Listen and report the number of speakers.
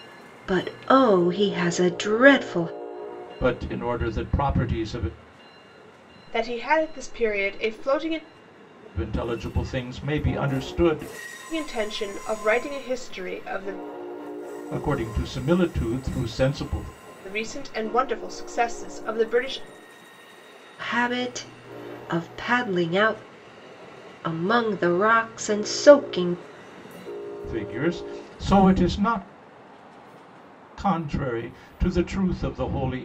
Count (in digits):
3